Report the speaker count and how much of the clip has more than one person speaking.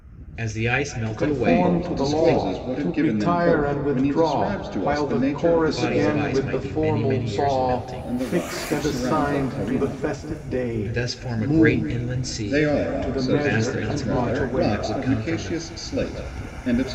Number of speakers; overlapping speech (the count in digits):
3, about 79%